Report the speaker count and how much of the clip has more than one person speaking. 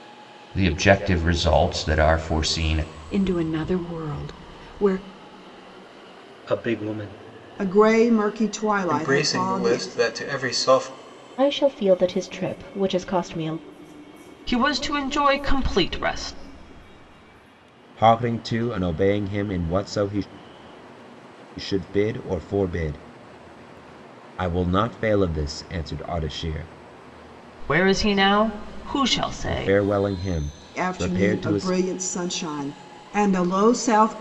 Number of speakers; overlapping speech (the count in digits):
8, about 7%